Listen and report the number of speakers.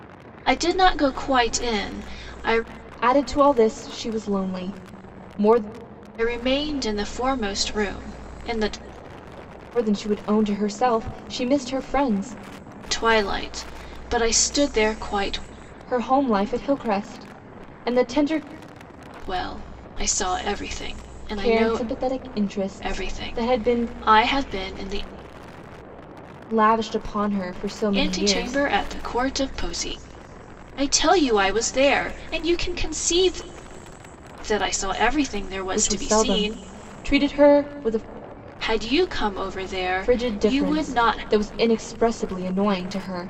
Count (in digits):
2